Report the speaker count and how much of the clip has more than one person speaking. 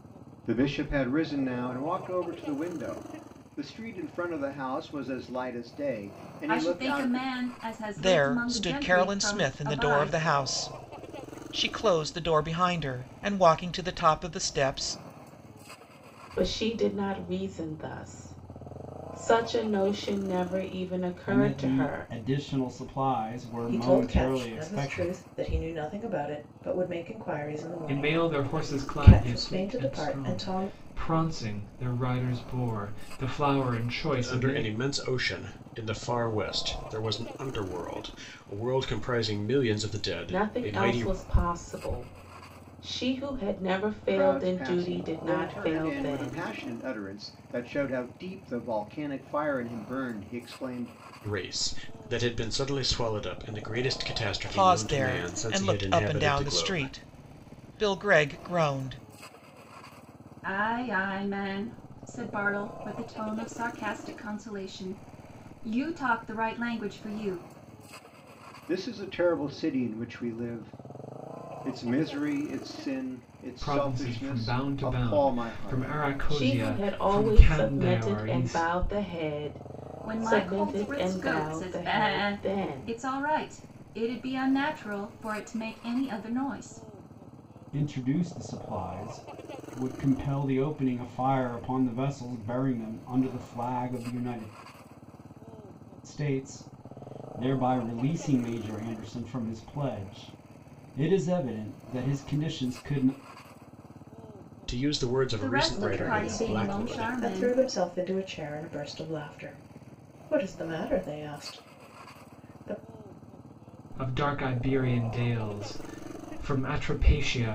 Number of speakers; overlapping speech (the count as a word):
eight, about 21%